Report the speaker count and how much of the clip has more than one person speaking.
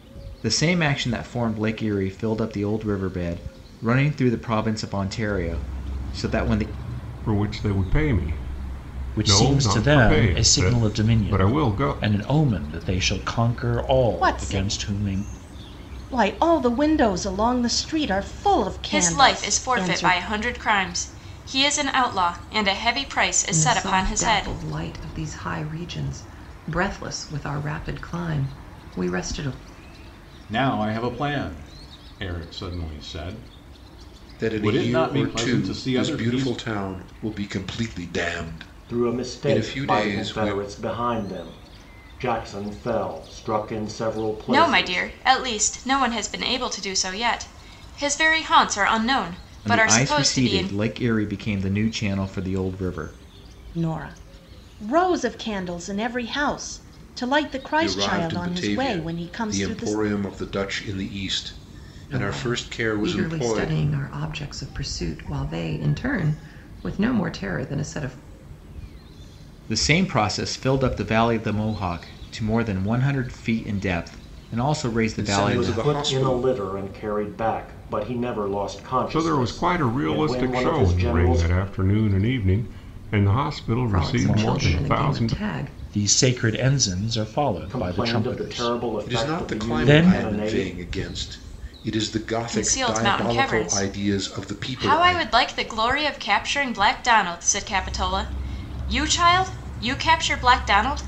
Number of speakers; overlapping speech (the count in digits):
9, about 28%